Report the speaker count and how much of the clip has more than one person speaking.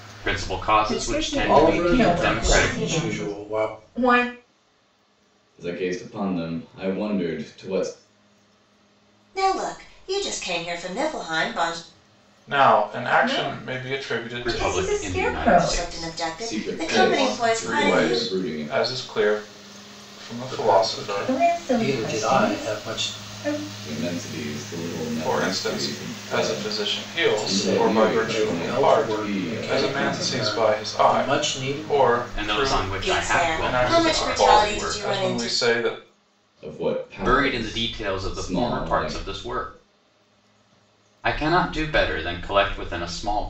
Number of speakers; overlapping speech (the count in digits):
7, about 53%